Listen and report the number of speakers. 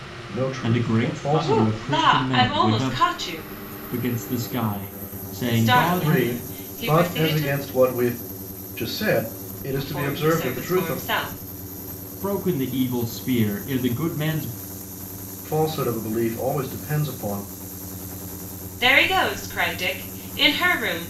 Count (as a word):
three